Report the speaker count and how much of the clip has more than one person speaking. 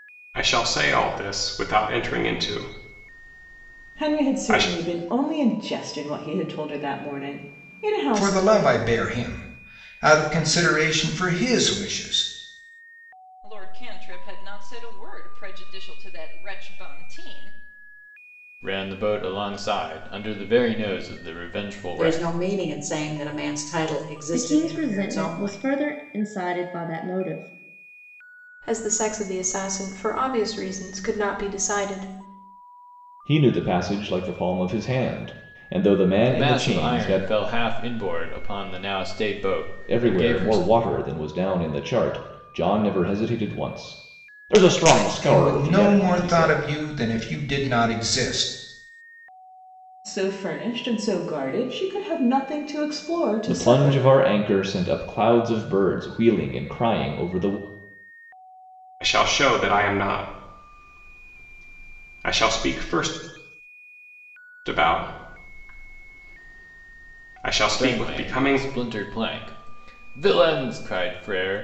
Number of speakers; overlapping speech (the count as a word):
nine, about 11%